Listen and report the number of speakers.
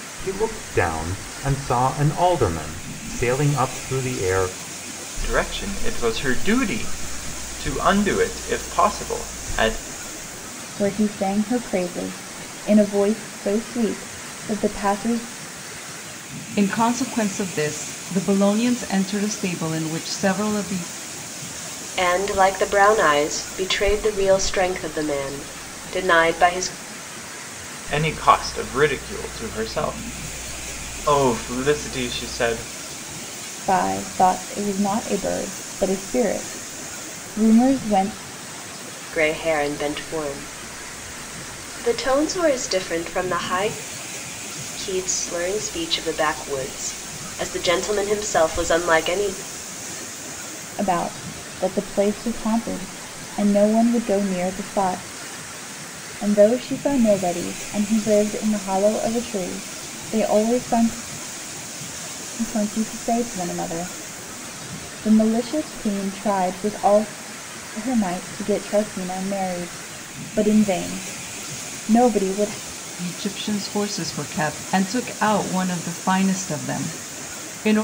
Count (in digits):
5